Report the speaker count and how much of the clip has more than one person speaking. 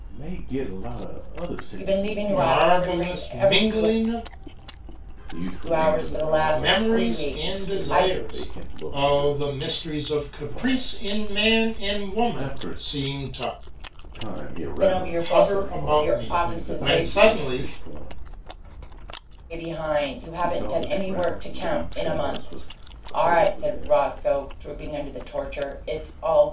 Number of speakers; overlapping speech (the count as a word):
three, about 54%